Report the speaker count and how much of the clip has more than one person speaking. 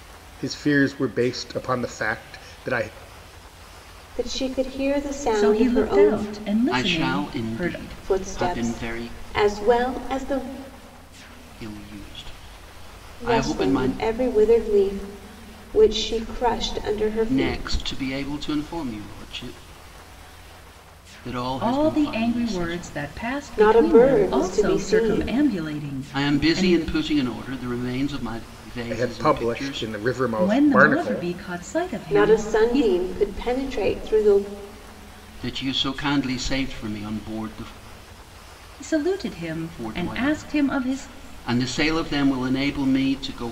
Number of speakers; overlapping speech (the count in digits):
4, about 29%